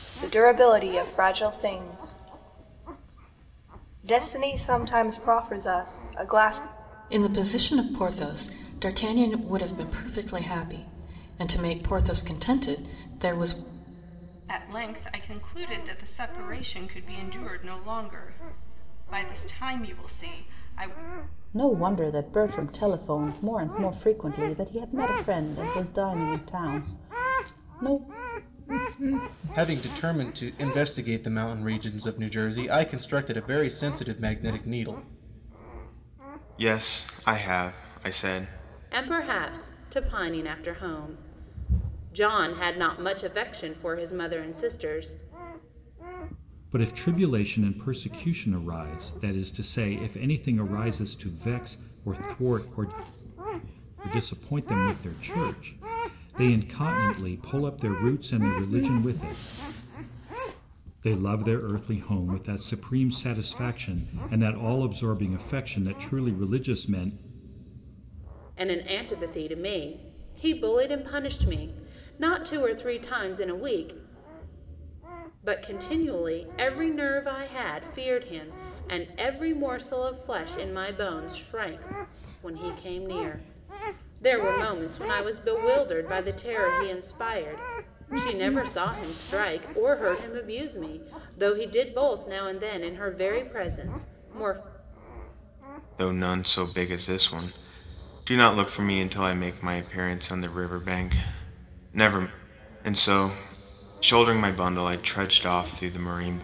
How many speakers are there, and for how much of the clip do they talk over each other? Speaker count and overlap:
eight, no overlap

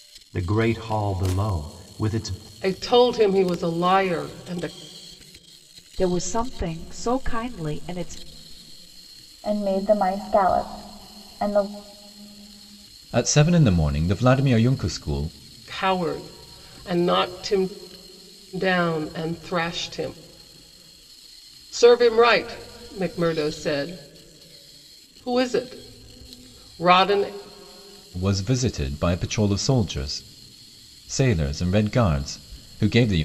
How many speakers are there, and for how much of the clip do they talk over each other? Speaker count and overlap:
five, no overlap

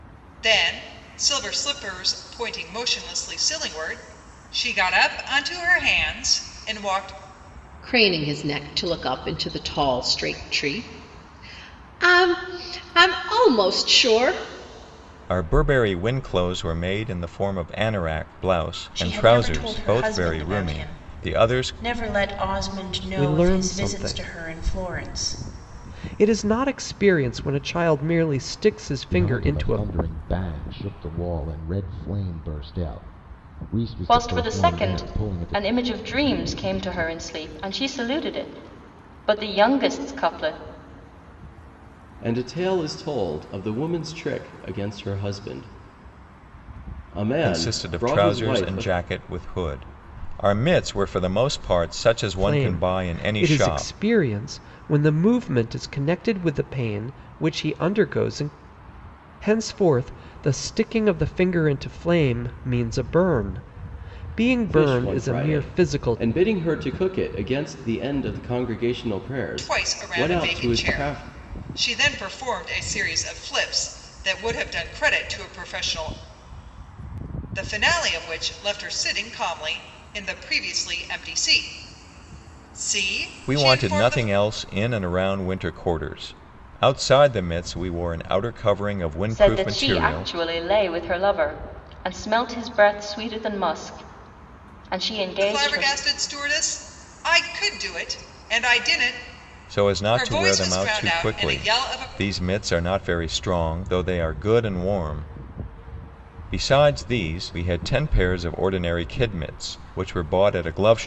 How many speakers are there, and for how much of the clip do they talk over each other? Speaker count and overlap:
eight, about 17%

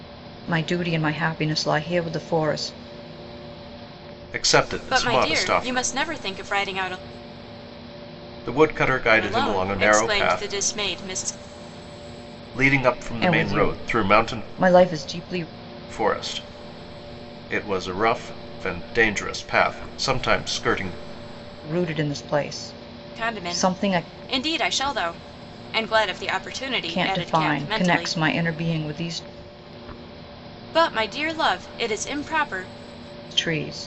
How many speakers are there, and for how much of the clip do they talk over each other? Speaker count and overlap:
three, about 18%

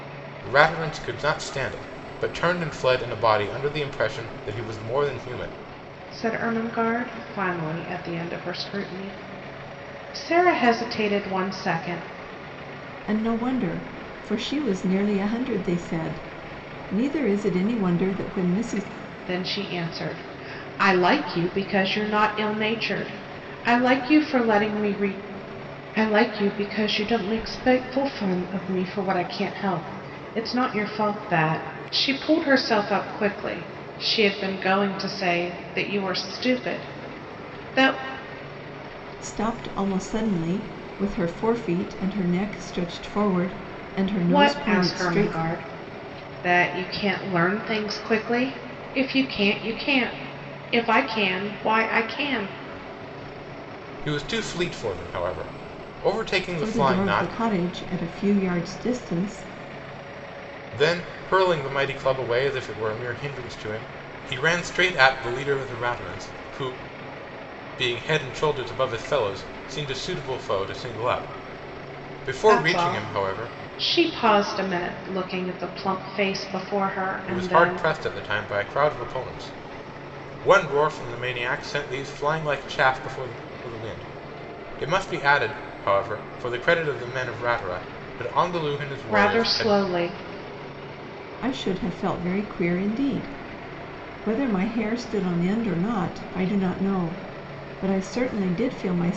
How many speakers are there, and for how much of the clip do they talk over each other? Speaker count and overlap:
three, about 5%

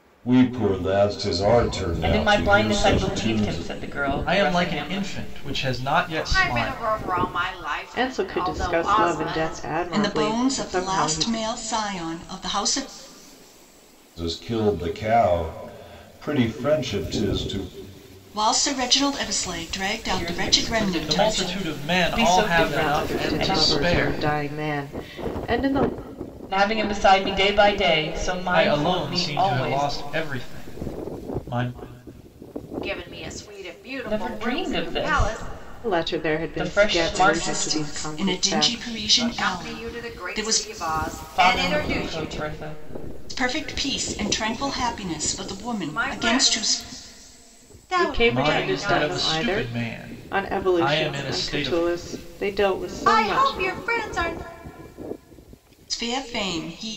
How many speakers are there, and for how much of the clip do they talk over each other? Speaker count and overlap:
six, about 45%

